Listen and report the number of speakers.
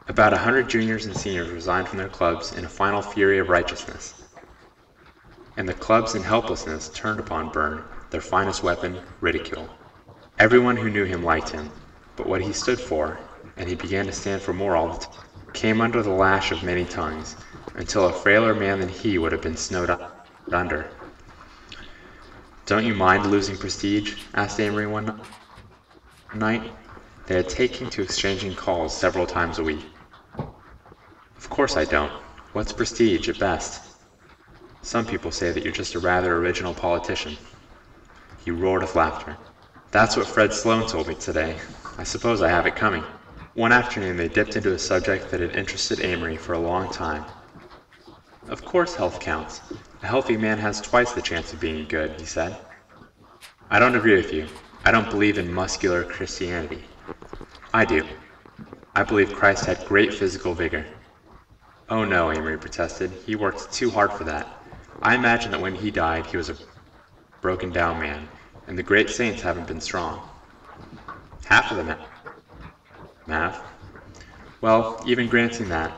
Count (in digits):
1